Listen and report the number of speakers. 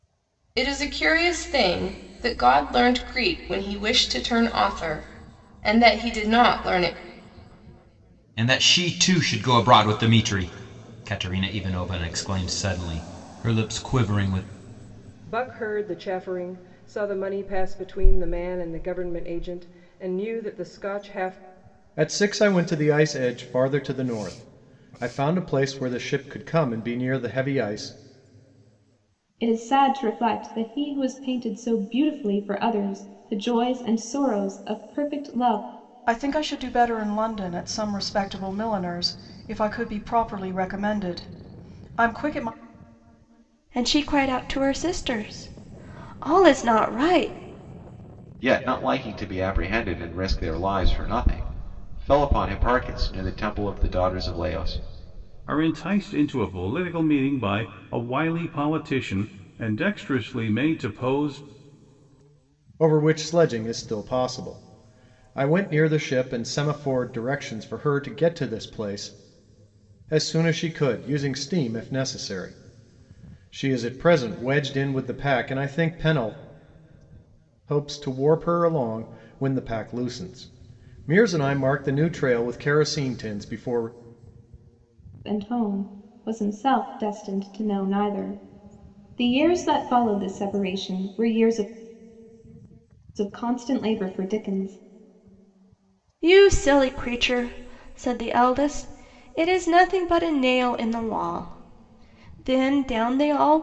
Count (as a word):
nine